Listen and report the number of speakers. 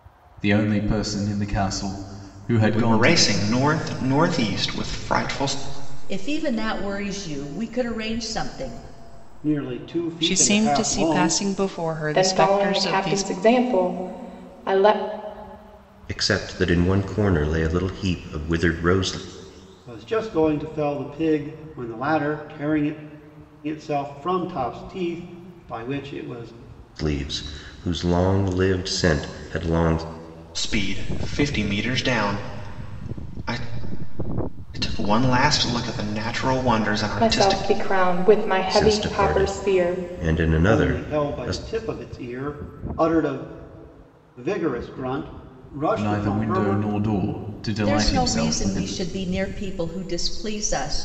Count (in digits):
7